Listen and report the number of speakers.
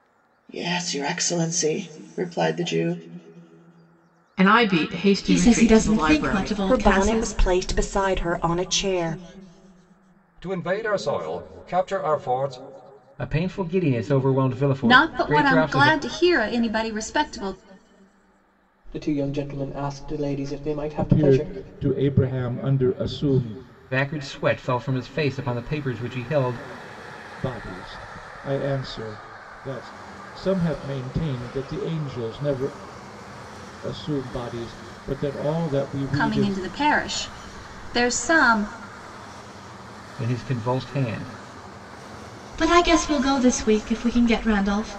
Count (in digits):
9